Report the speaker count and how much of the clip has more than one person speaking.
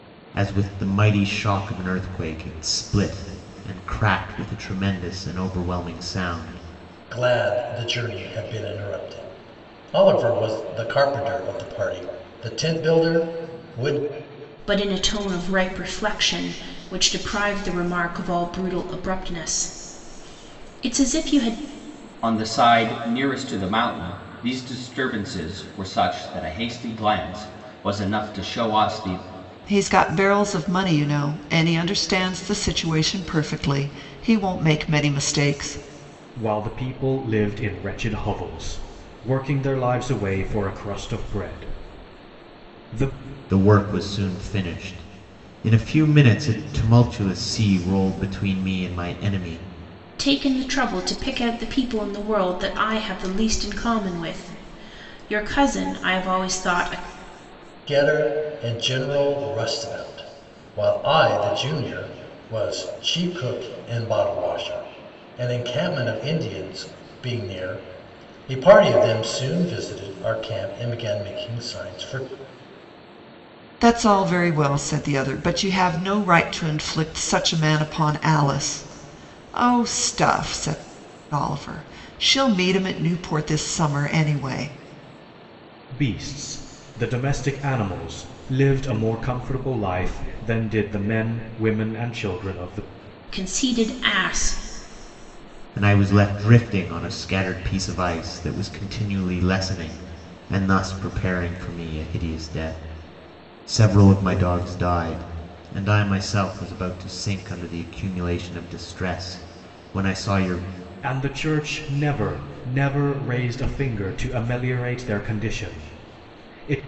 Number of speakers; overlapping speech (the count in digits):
6, no overlap